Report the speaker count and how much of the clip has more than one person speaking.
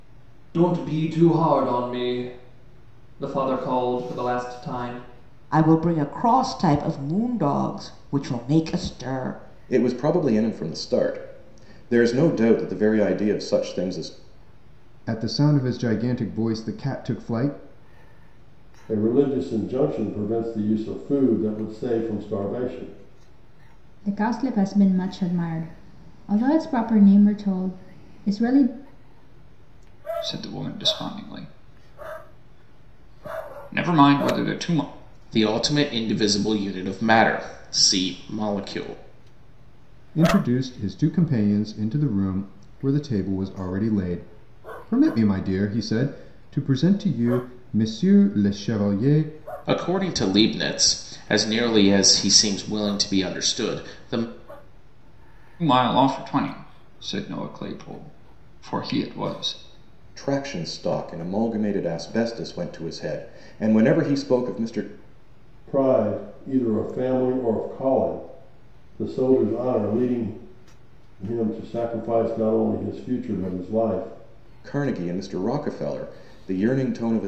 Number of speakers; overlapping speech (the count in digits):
8, no overlap